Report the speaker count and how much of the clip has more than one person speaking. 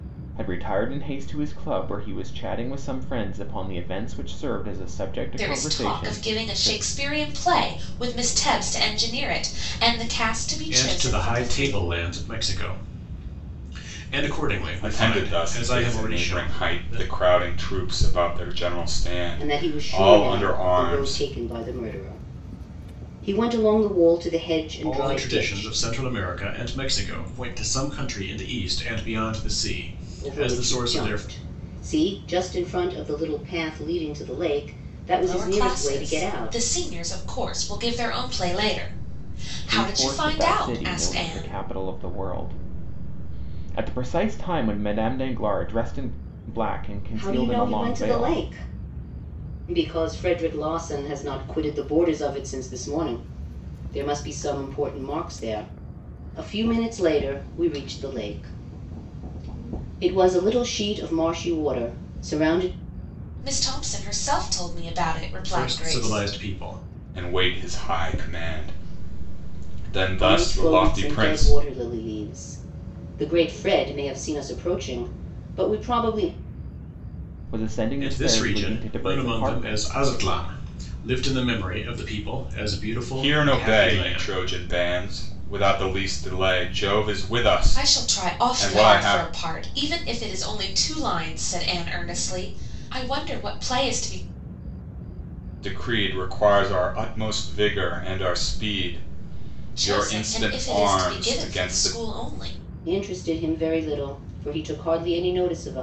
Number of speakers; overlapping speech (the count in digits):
5, about 22%